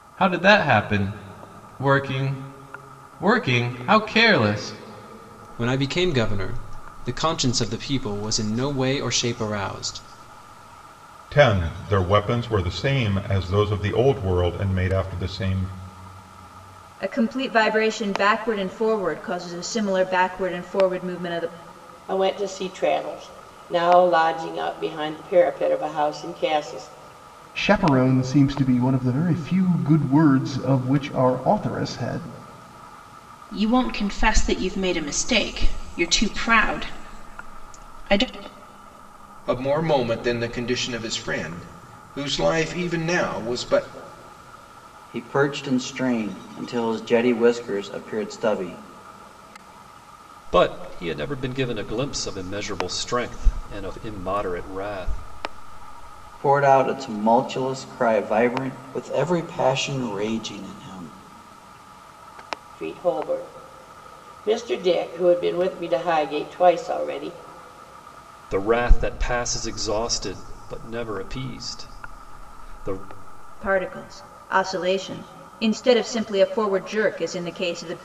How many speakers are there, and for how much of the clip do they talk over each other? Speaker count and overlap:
10, no overlap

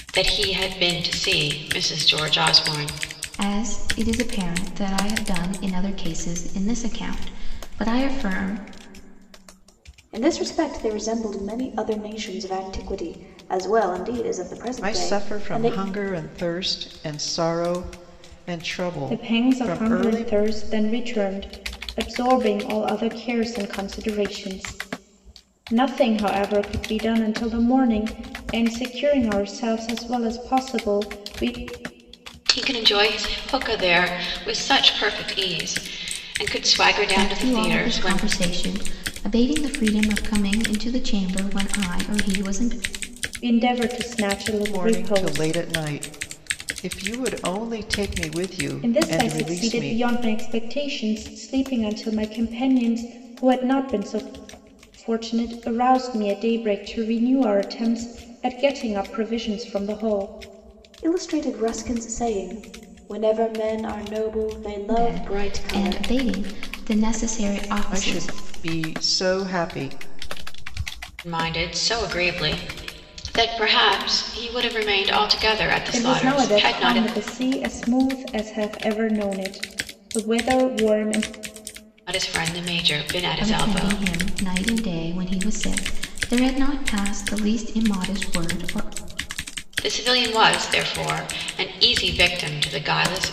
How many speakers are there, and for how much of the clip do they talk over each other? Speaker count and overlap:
5, about 10%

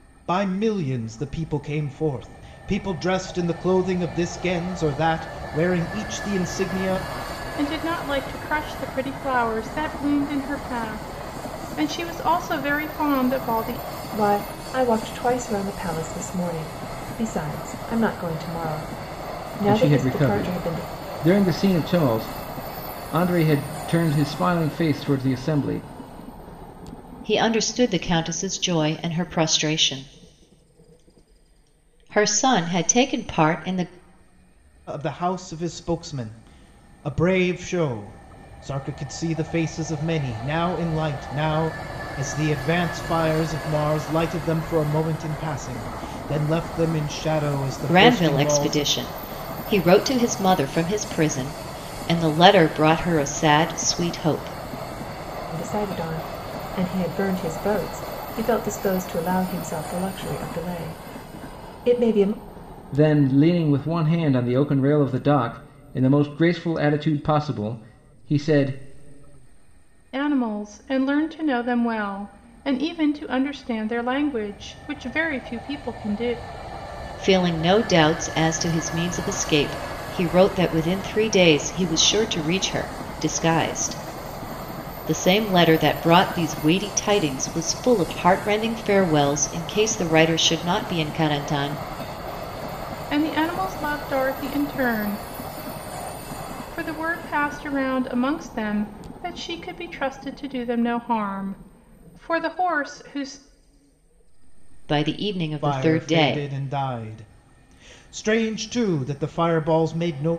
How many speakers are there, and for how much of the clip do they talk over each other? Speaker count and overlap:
5, about 3%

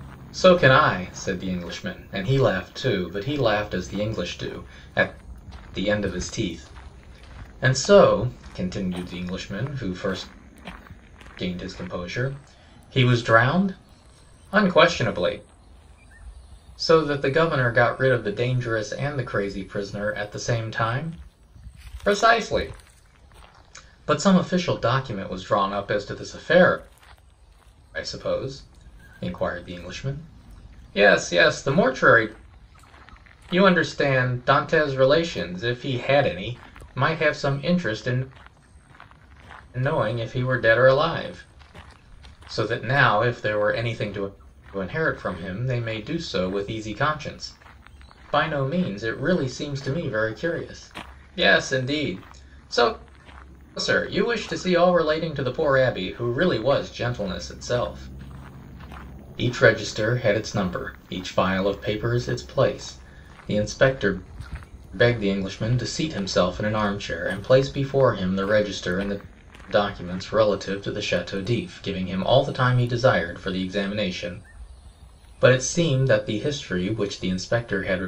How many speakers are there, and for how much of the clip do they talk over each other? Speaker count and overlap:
1, no overlap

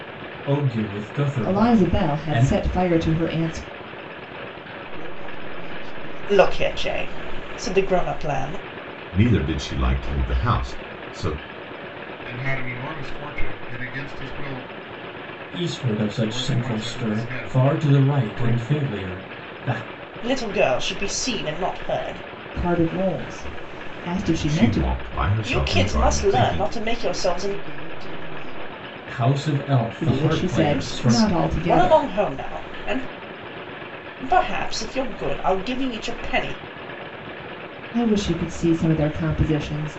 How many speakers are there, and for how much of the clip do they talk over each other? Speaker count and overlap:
6, about 22%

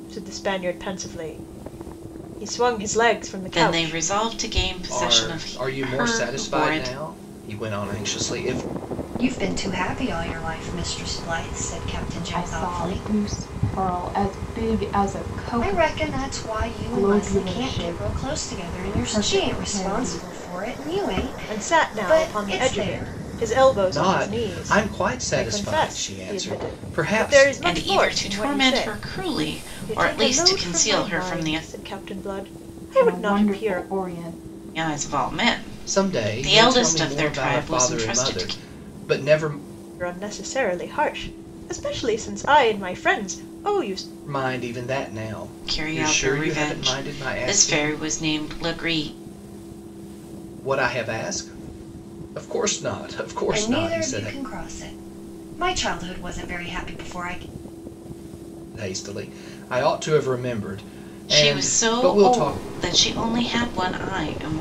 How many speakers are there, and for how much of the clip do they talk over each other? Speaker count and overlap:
5, about 36%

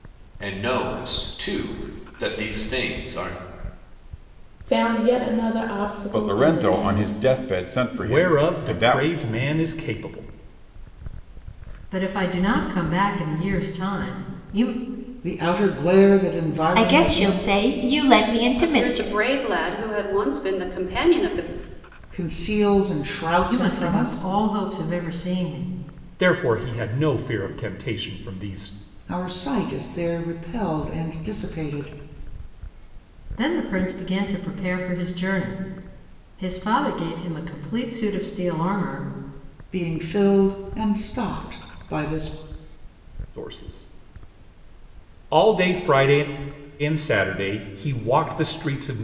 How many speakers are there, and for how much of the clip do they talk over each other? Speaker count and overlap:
8, about 9%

